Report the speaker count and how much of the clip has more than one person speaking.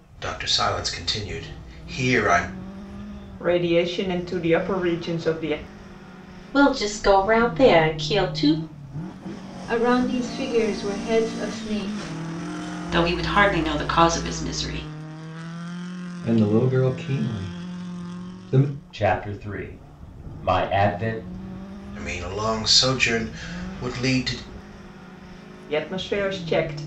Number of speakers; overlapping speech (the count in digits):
7, no overlap